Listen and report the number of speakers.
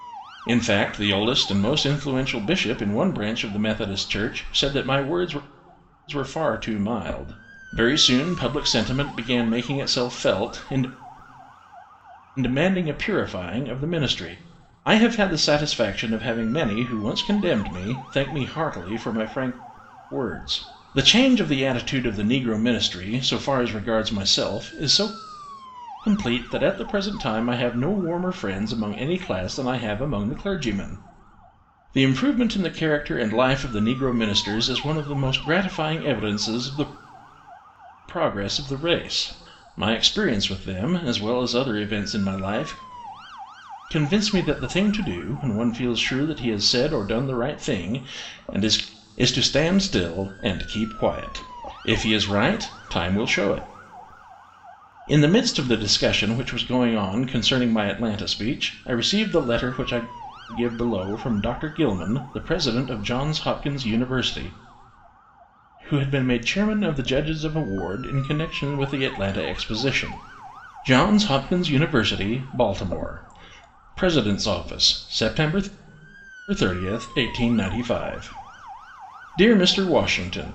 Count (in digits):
1